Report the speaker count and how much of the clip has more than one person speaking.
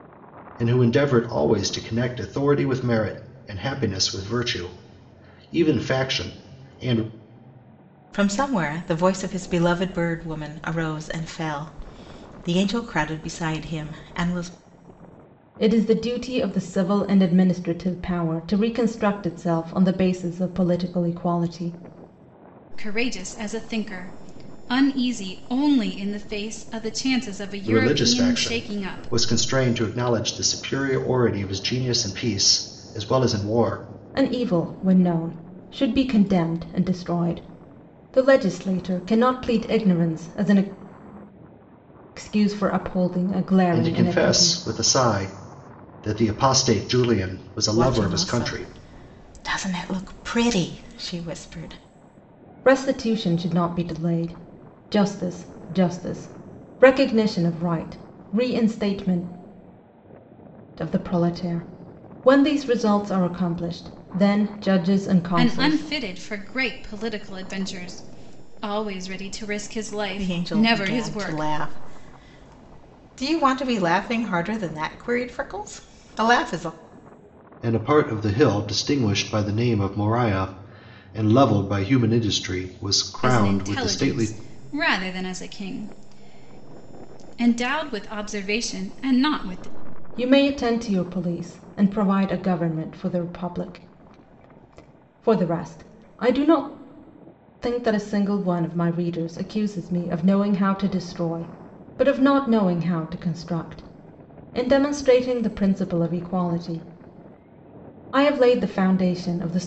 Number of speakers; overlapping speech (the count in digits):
4, about 6%